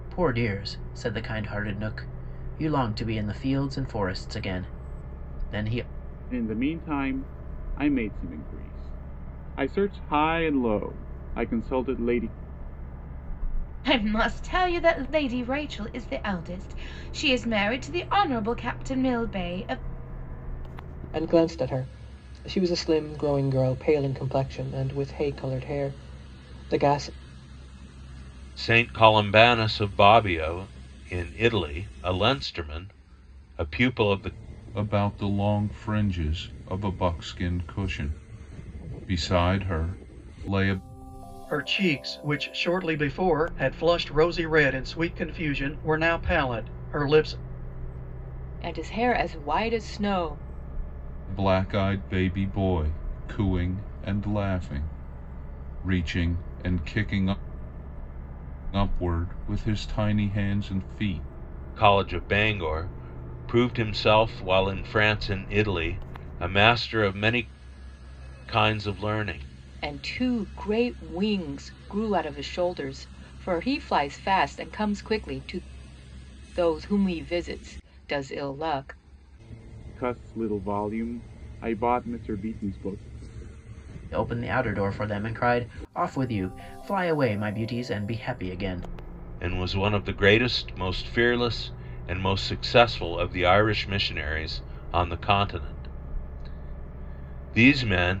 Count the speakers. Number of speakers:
8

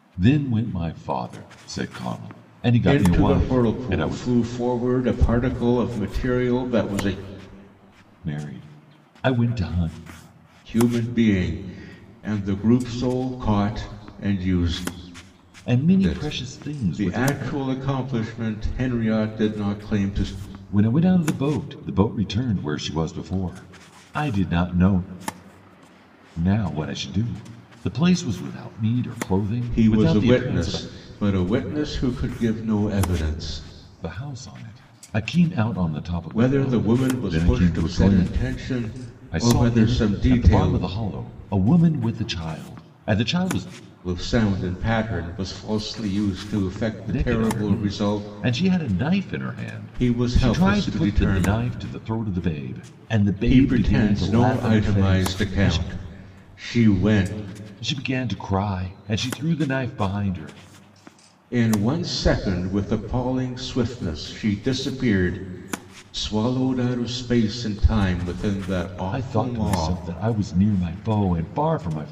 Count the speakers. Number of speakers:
2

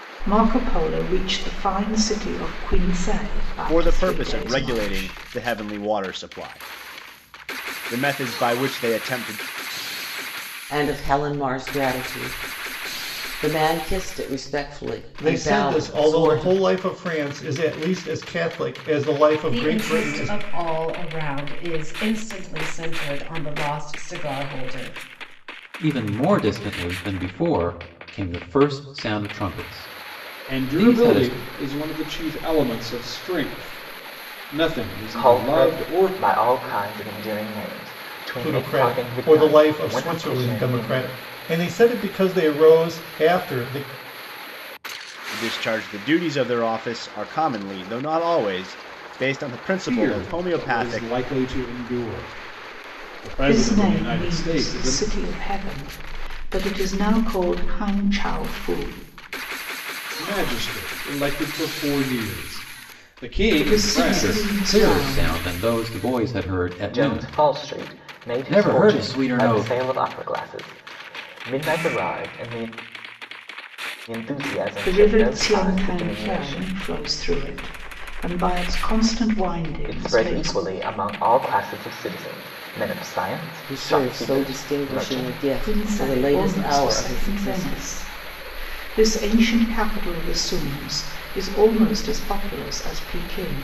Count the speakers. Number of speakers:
8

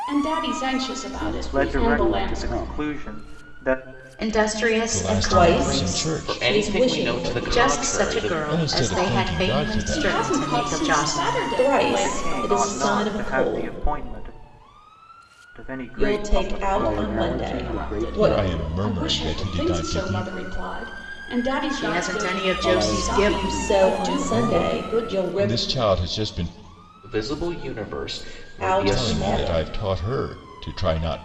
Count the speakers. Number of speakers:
7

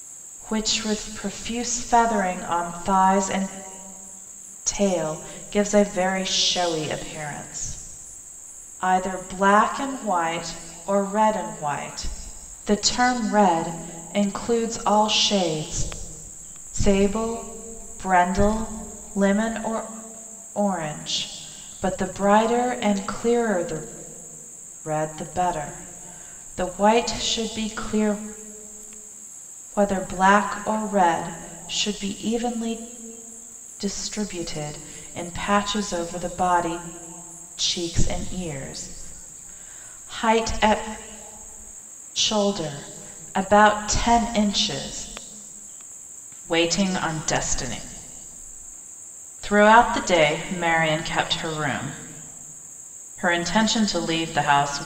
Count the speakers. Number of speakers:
1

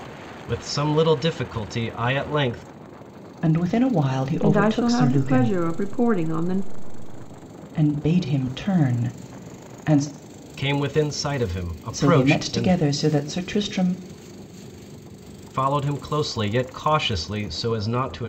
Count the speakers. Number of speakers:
3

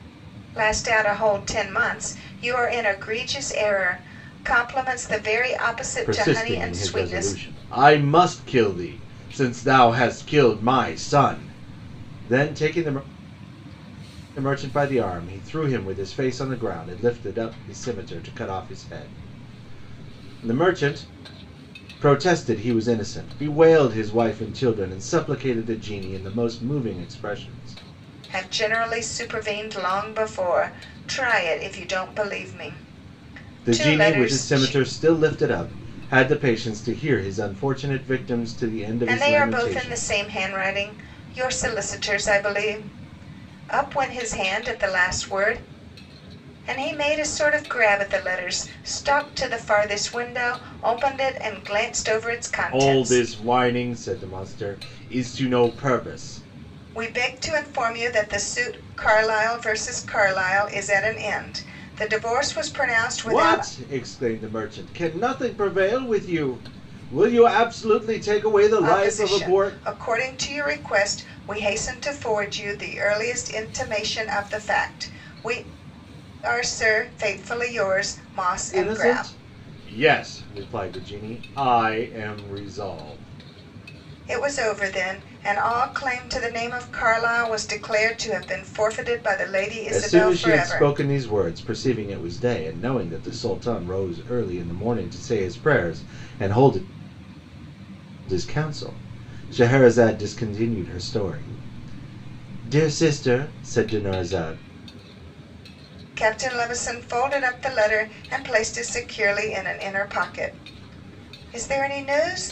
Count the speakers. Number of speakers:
2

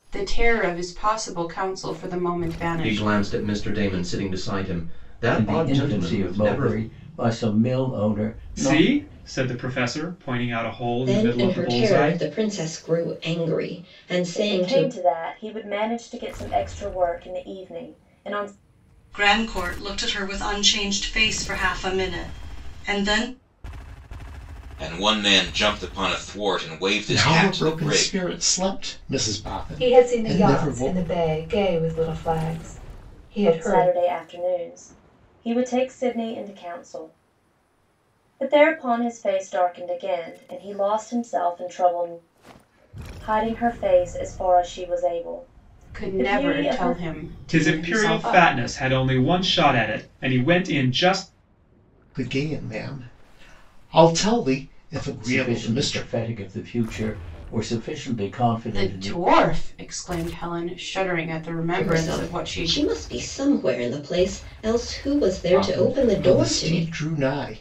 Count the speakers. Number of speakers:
10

